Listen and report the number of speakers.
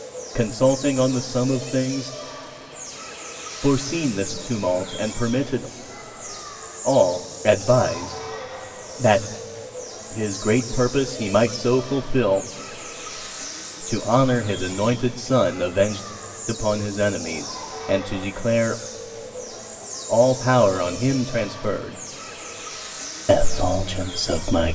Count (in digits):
1